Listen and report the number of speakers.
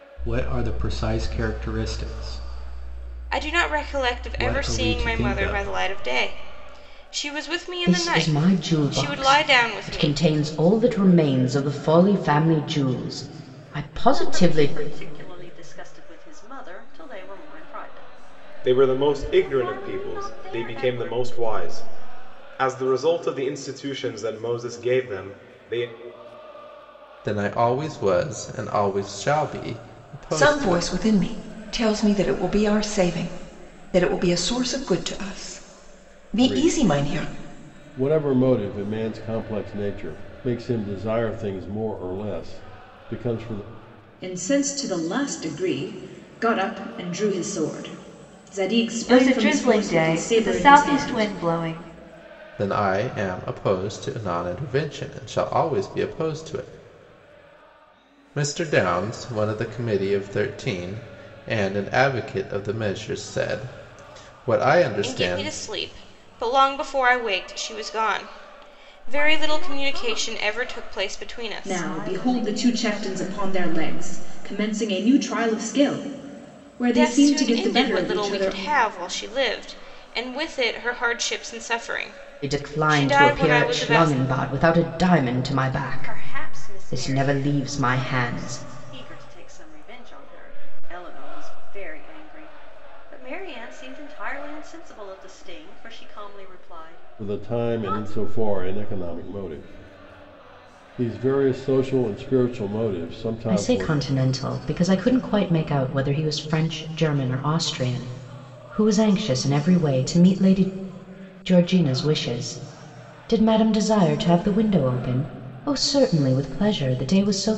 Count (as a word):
ten